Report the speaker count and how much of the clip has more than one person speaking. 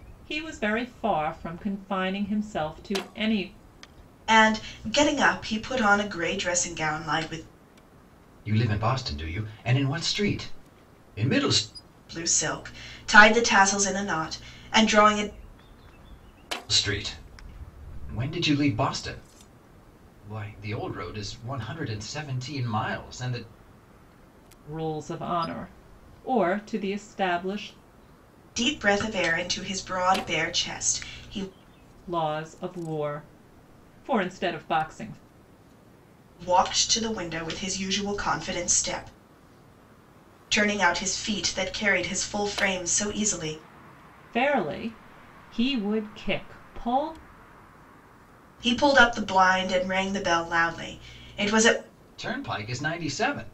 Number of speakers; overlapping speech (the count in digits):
3, no overlap